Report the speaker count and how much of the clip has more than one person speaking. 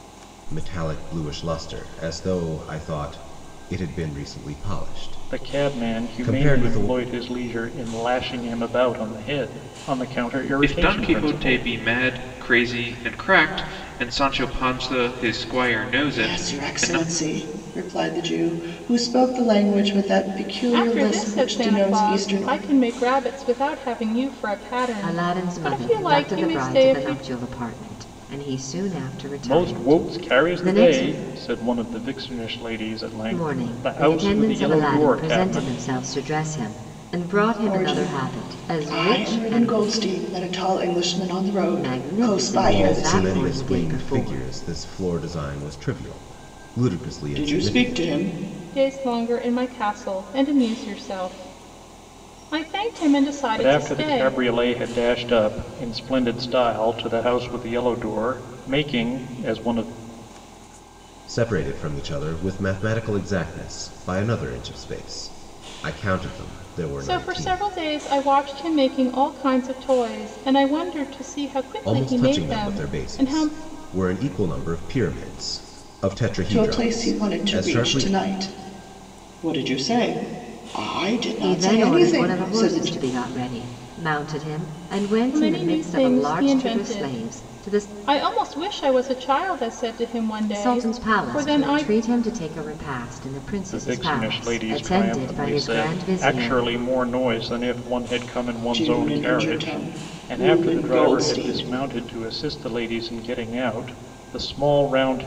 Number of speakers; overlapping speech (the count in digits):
6, about 32%